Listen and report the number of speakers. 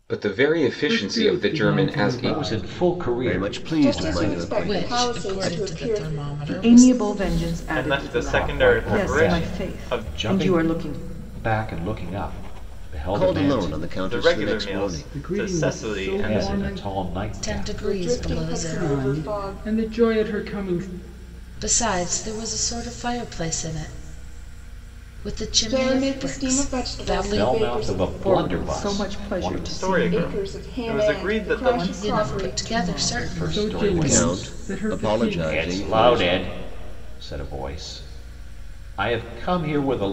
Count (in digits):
8